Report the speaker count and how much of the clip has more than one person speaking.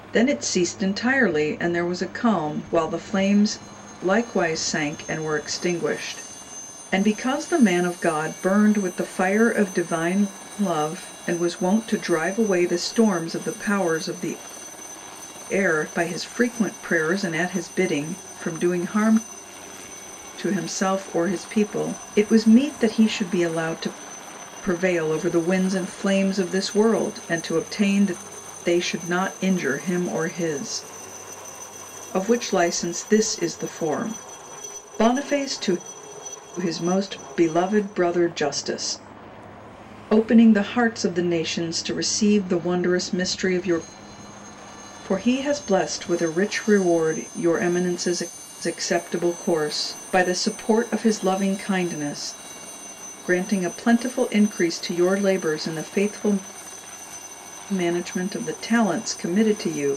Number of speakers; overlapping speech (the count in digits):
1, no overlap